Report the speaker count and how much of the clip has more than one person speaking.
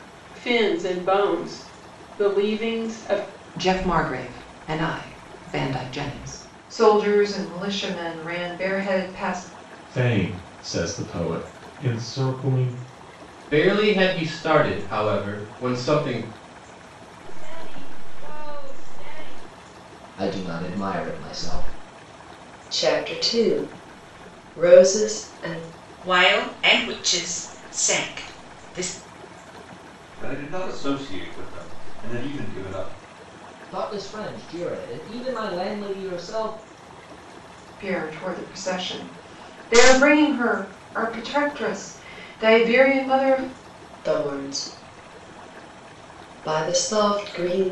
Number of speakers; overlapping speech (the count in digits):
10, no overlap